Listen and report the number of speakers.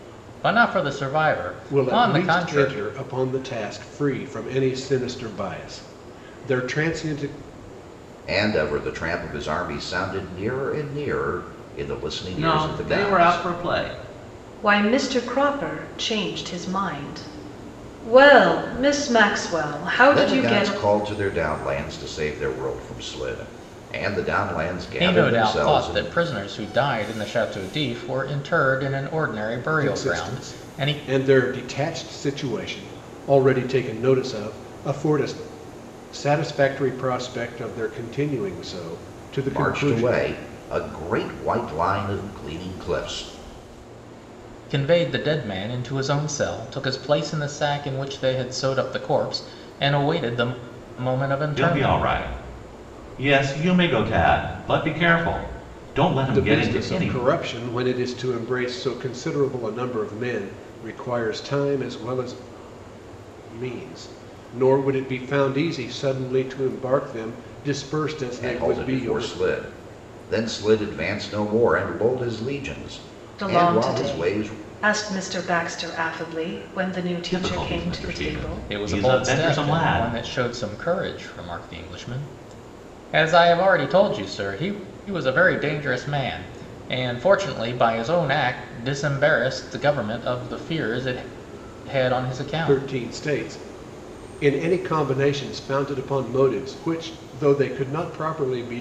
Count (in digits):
5